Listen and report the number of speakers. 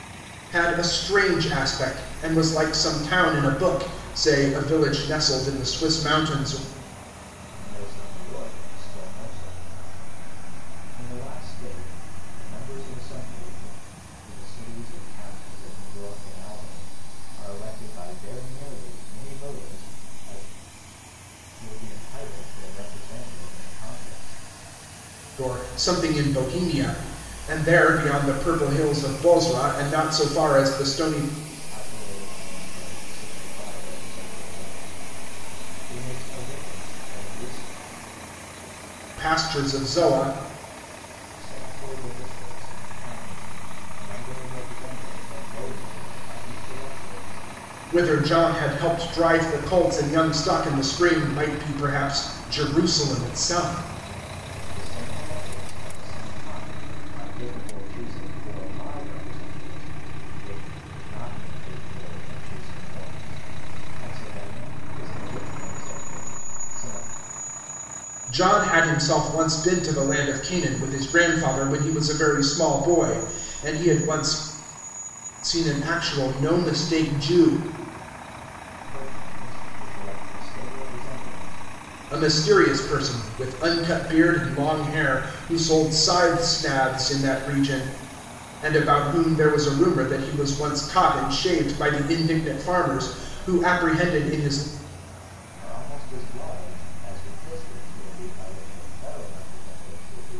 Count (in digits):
2